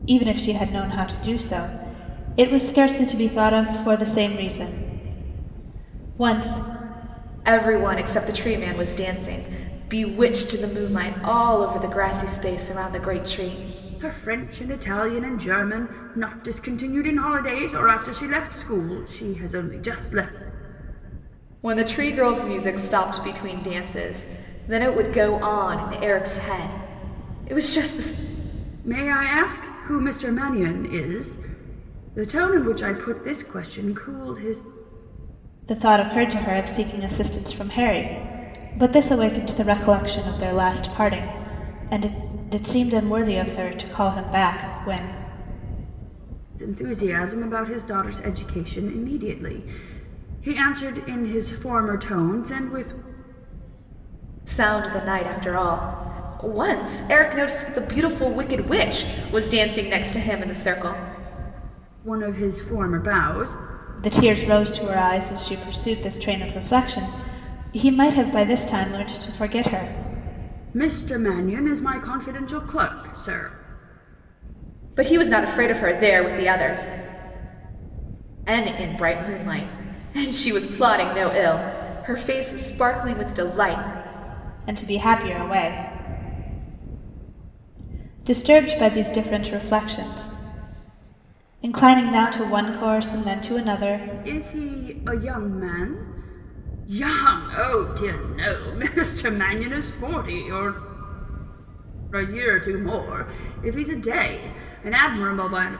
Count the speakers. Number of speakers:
3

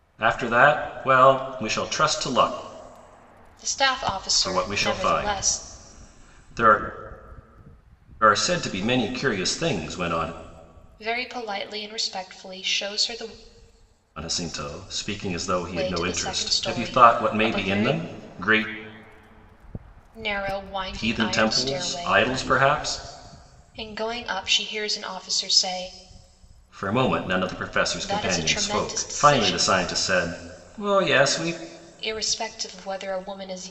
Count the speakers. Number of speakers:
2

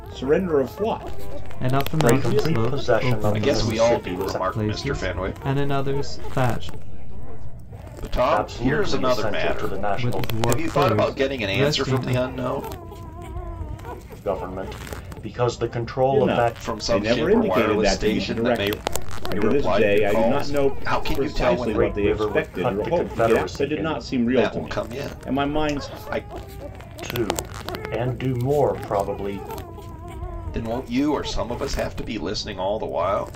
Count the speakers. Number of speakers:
5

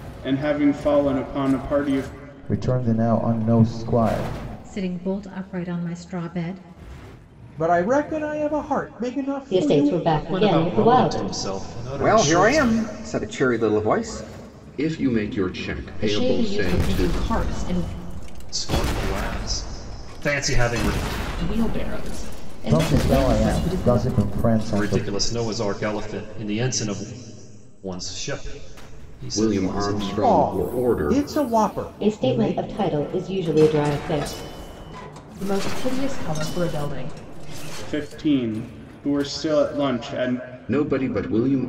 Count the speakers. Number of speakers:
9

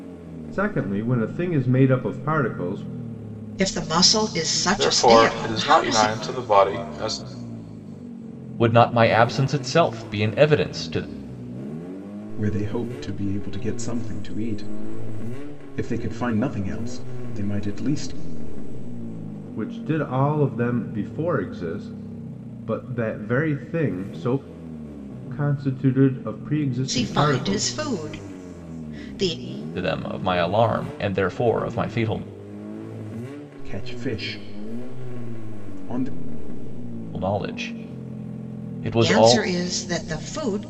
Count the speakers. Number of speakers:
5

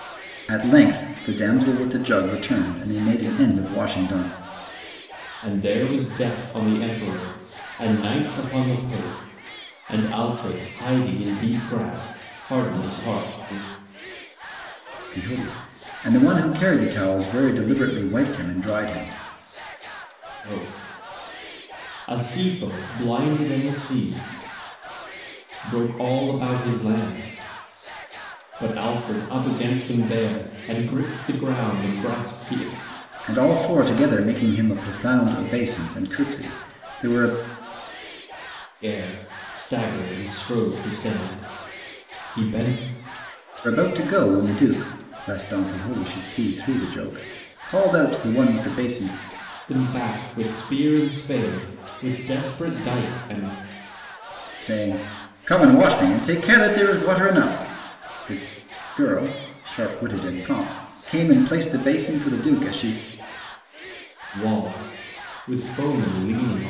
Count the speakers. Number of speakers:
2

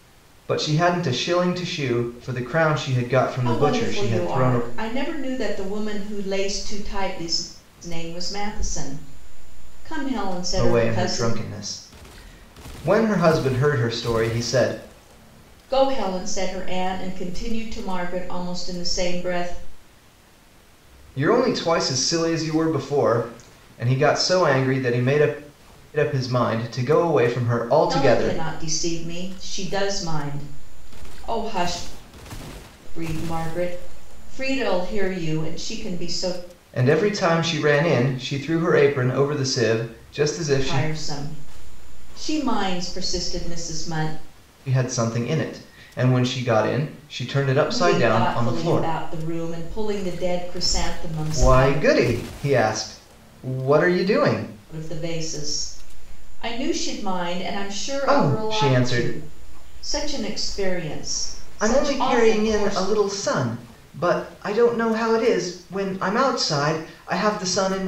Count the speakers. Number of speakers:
2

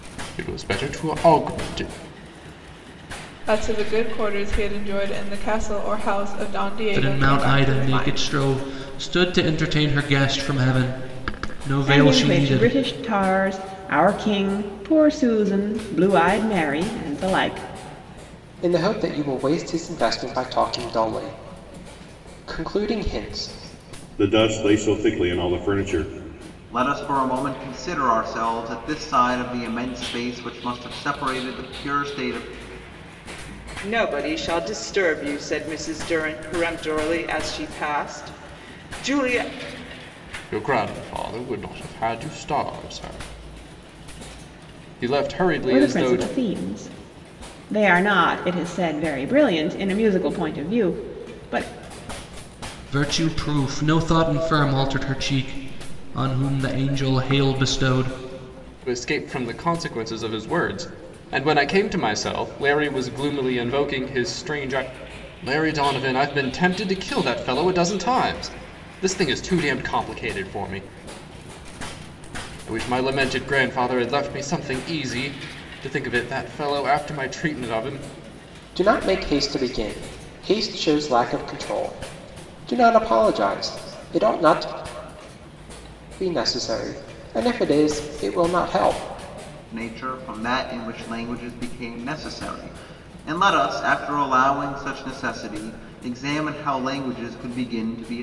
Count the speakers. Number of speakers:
8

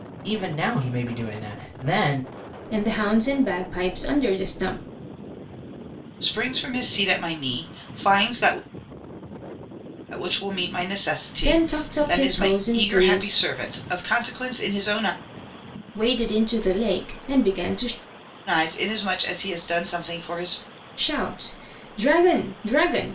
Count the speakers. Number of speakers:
3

